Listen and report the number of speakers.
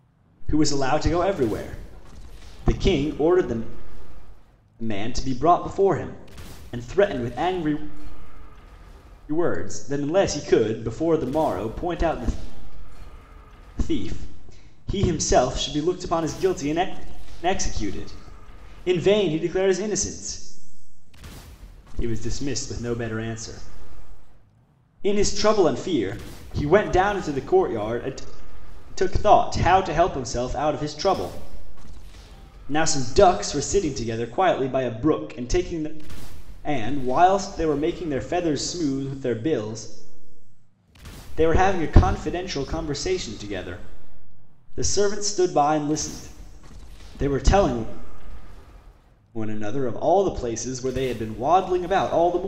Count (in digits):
1